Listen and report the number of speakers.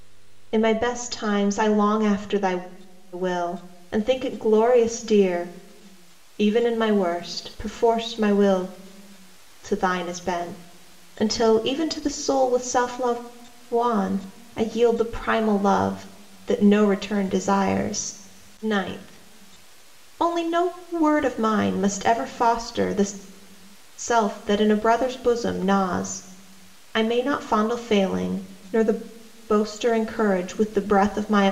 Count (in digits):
1